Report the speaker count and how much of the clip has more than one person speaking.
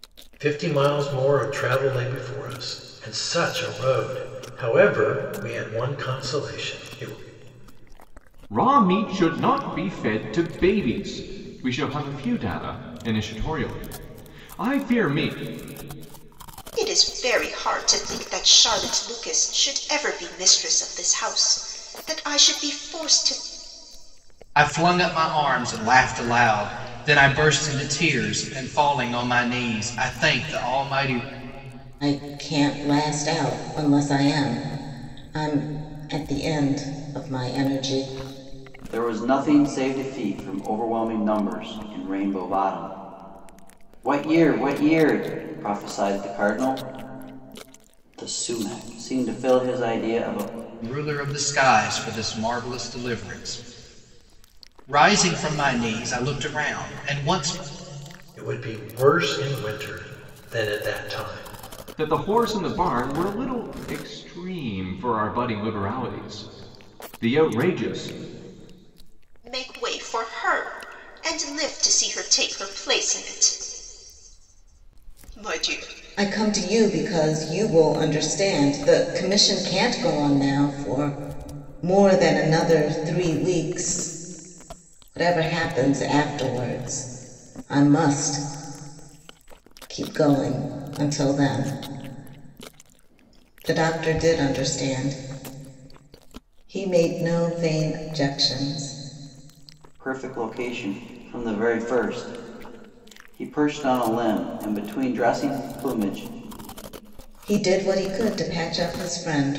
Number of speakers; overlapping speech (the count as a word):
six, no overlap